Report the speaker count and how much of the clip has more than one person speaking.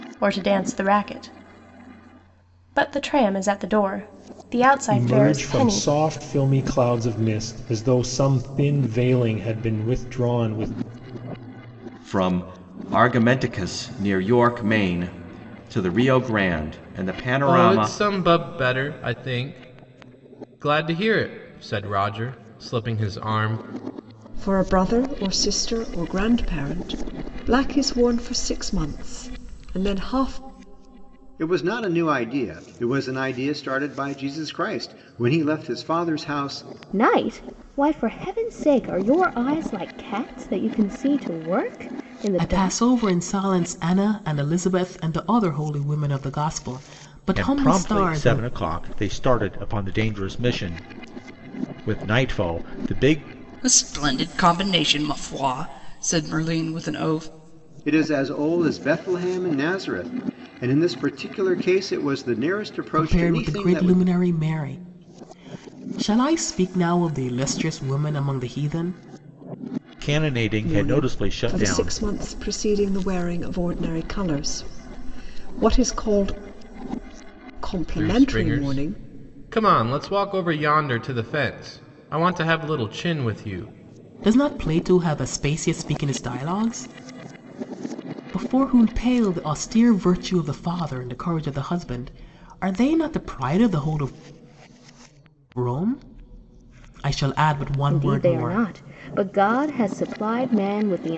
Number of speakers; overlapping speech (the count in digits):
10, about 8%